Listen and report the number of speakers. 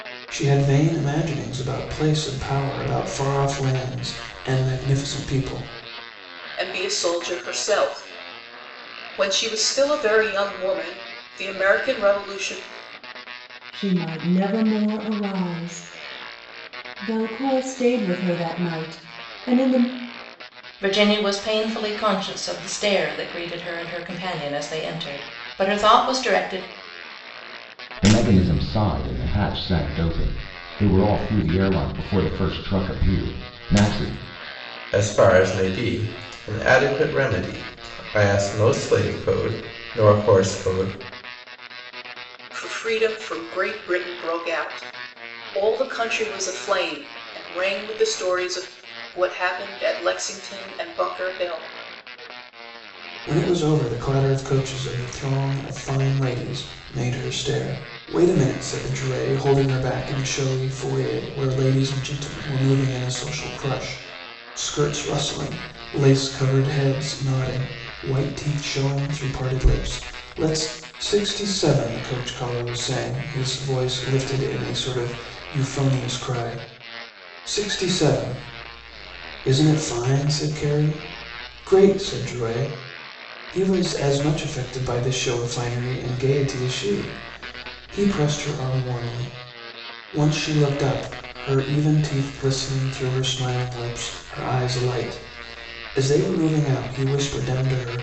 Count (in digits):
6